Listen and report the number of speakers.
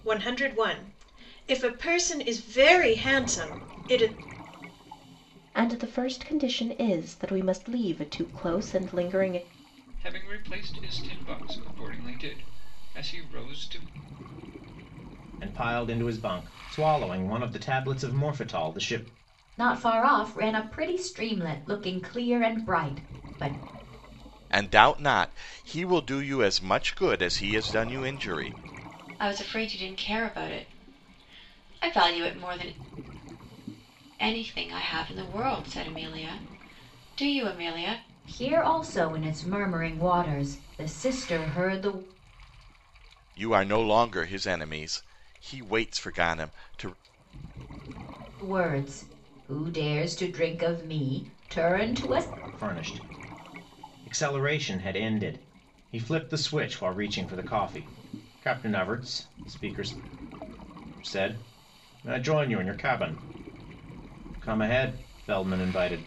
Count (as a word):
seven